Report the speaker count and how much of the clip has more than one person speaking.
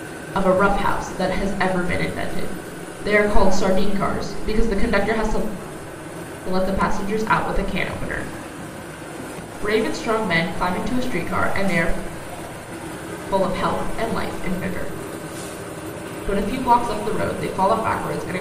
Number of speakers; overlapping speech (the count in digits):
1, no overlap